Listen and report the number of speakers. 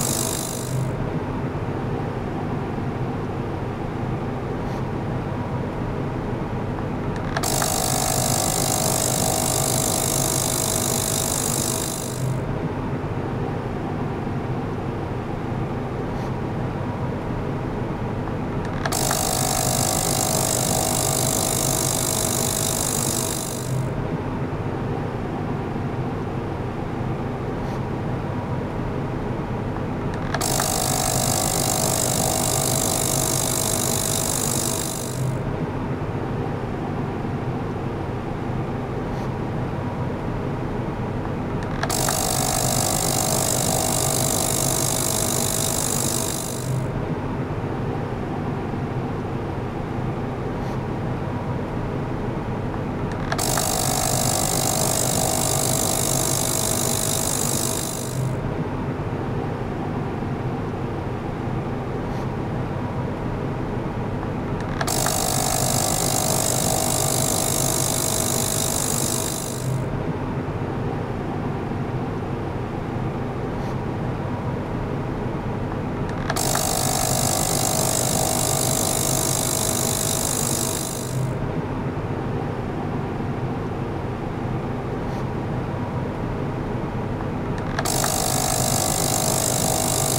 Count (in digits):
0